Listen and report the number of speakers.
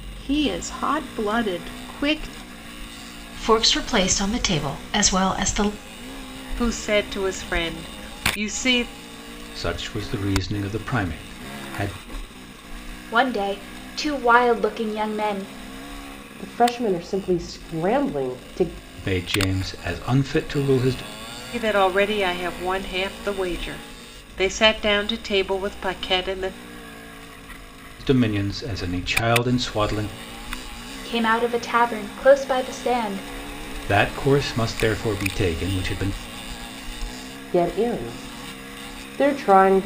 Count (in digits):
6